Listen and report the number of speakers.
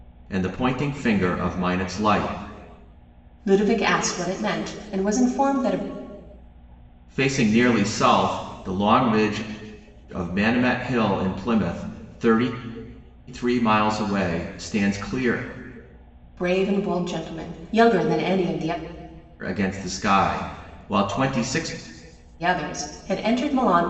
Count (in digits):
2